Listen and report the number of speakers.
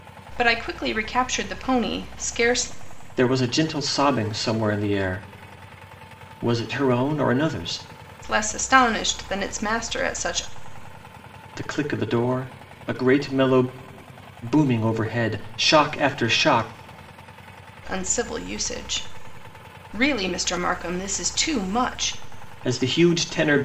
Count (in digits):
2